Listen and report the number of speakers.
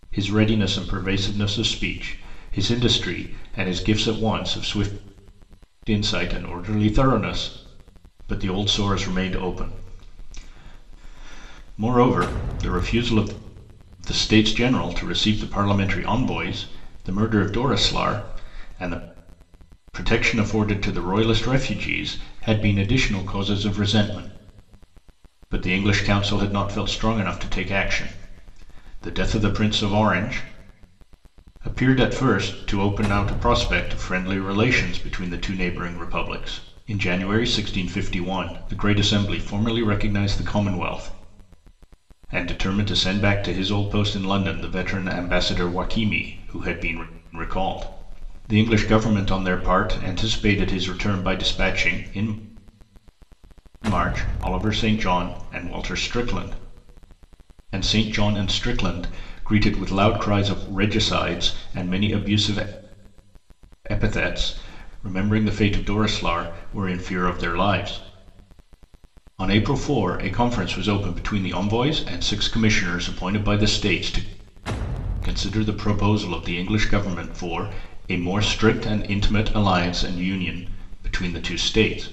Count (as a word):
one